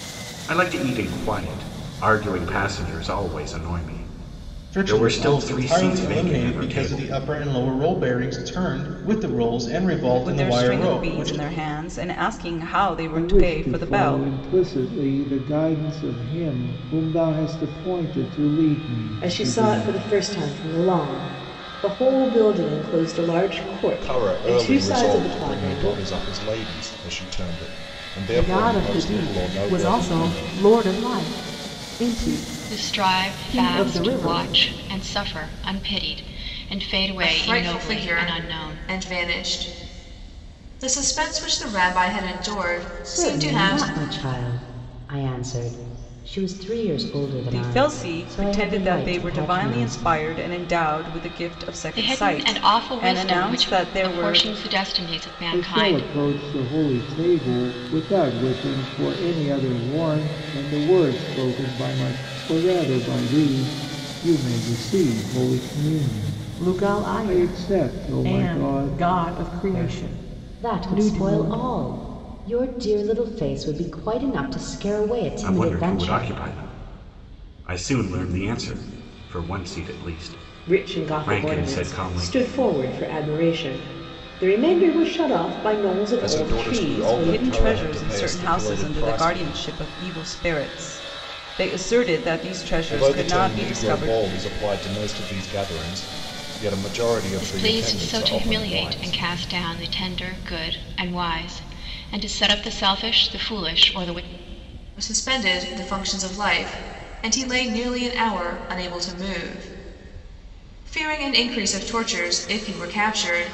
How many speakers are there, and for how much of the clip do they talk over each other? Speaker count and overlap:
10, about 30%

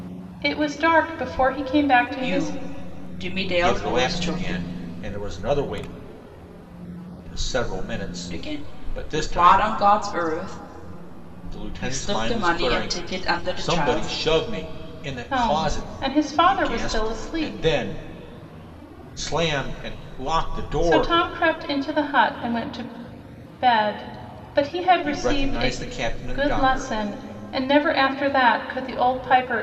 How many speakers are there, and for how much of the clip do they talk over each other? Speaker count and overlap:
3, about 29%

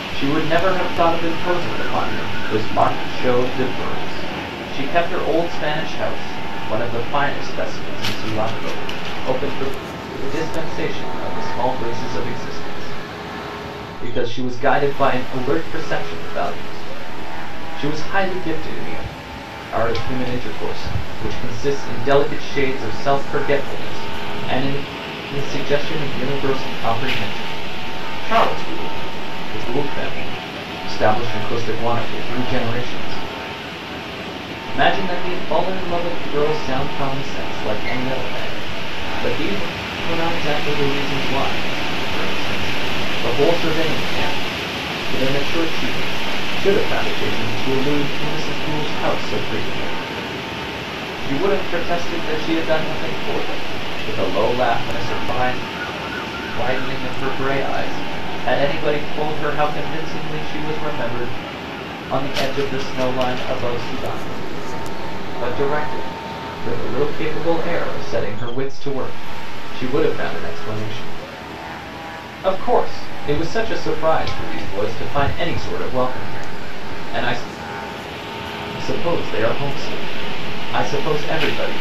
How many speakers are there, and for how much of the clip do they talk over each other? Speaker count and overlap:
1, no overlap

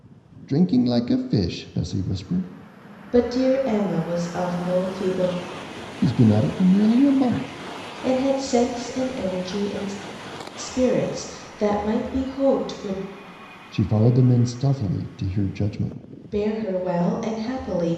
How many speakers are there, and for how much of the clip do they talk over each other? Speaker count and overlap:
2, no overlap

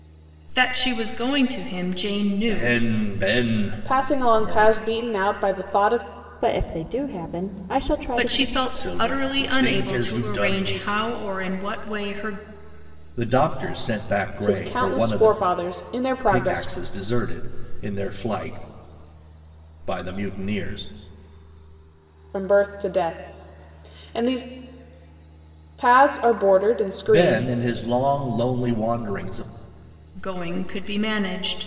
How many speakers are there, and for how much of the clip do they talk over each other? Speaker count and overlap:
4, about 19%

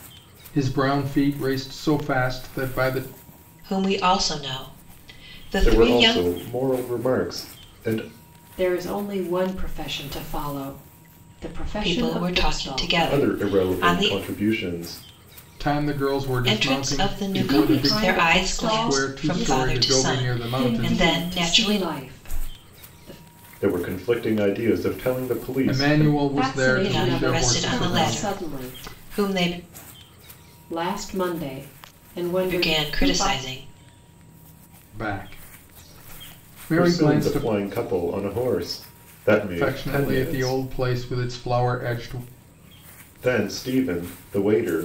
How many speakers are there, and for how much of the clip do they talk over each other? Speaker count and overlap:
4, about 32%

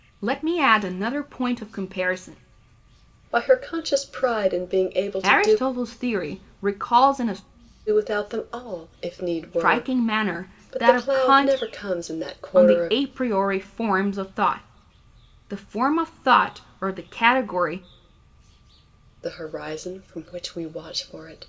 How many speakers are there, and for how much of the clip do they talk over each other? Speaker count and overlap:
2, about 11%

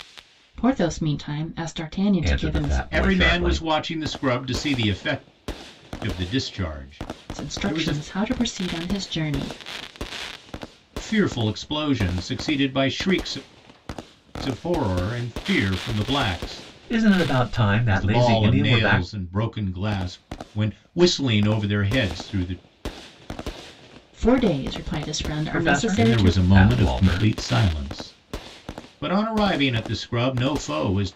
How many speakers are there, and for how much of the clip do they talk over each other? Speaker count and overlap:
3, about 16%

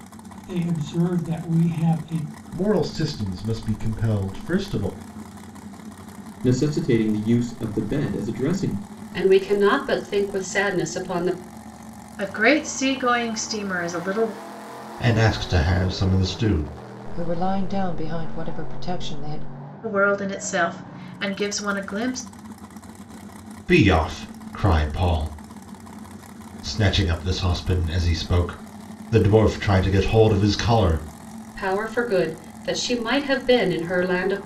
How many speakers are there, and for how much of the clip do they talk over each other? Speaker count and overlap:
7, no overlap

